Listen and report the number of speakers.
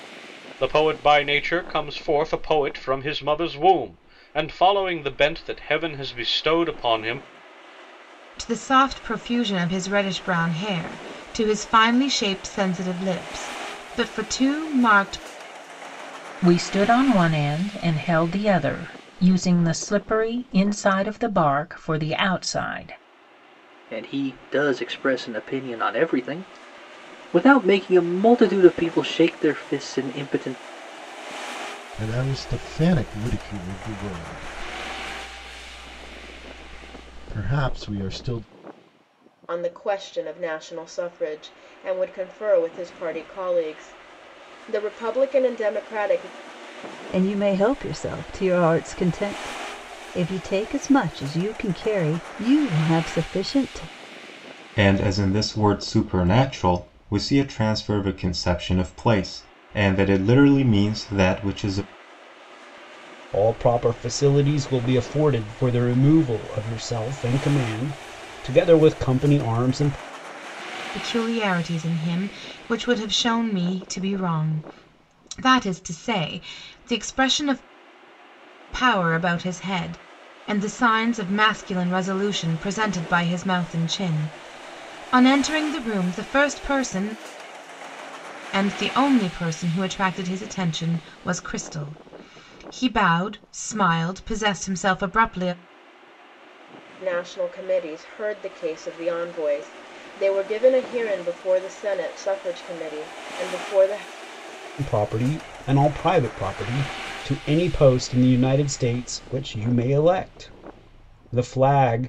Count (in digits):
9